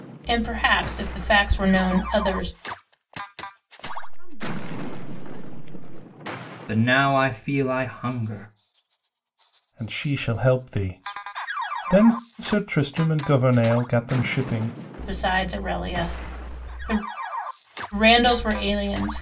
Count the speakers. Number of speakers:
4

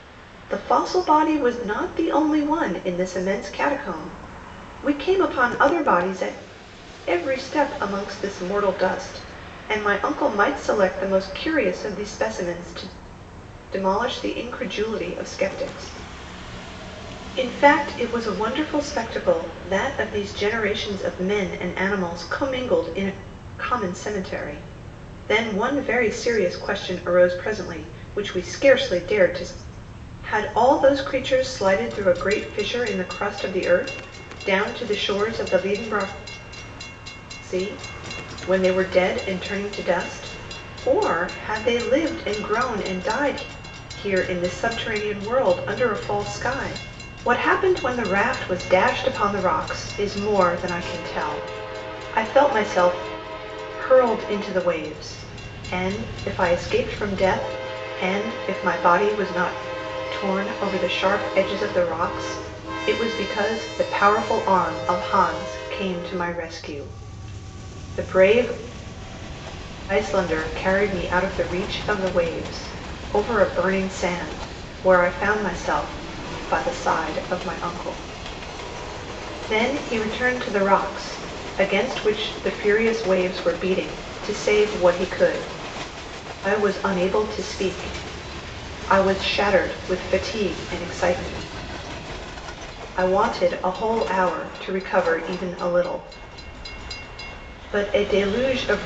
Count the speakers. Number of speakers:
1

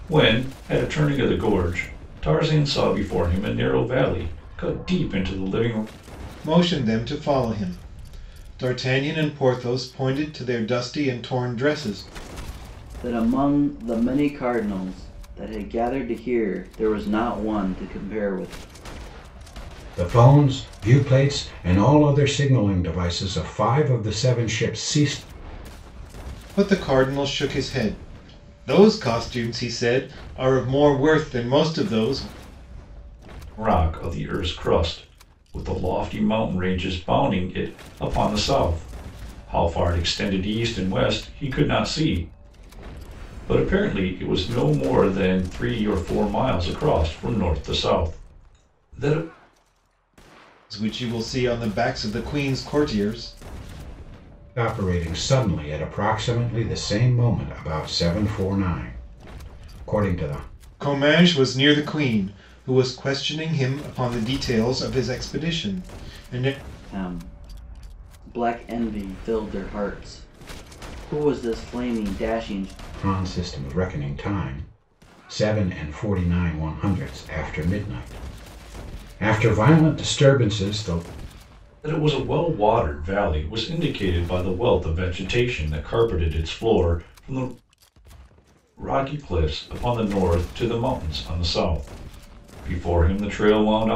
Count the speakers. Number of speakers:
4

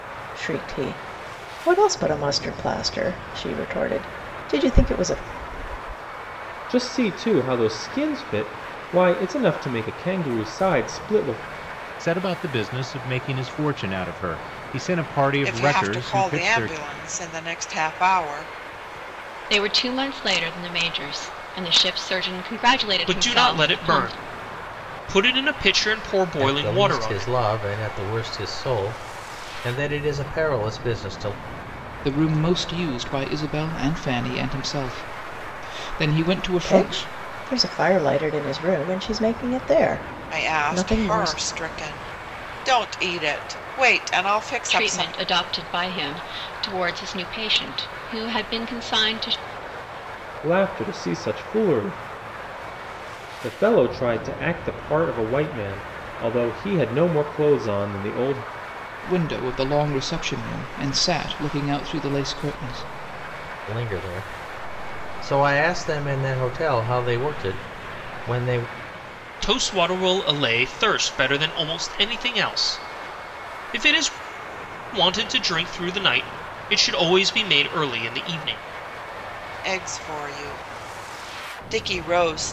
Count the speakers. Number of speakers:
8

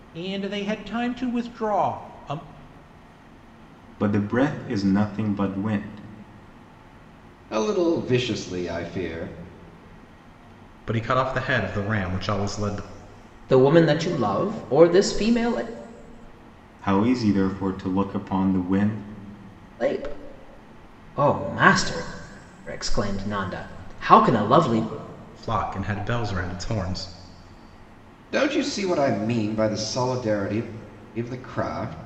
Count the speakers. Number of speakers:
5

